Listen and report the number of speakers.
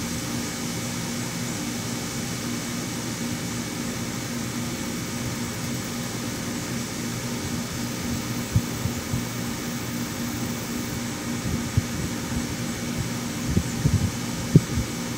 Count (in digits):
0